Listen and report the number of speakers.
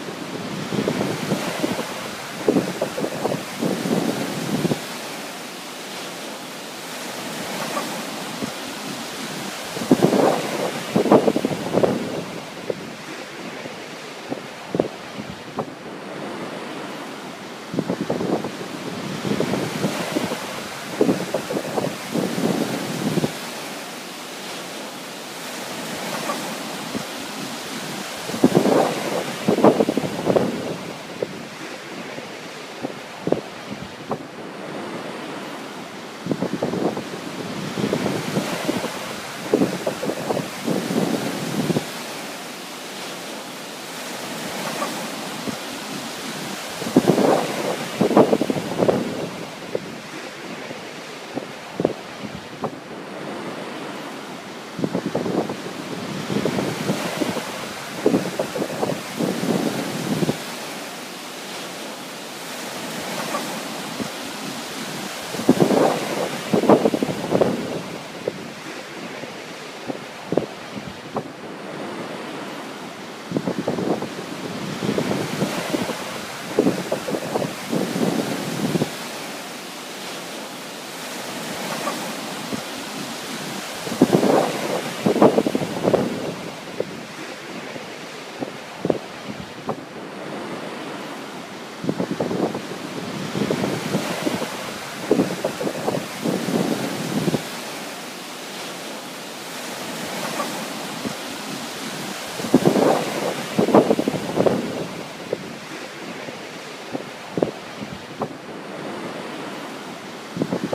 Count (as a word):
zero